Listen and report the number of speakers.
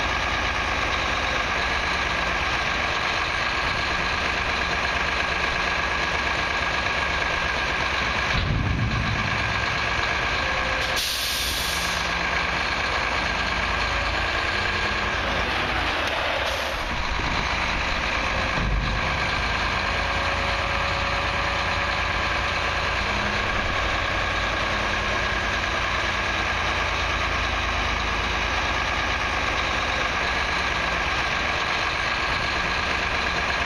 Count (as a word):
zero